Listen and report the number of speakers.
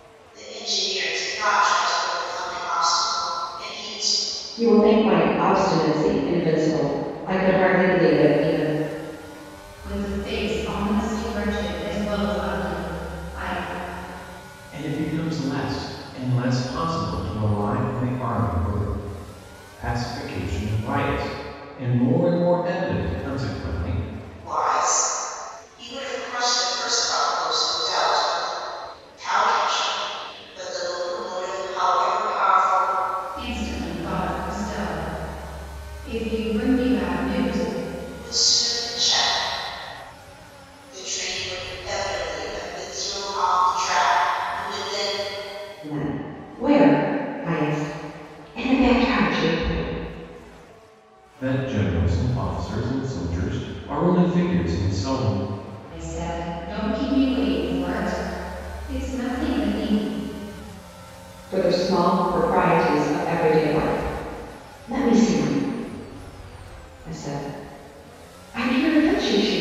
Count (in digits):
4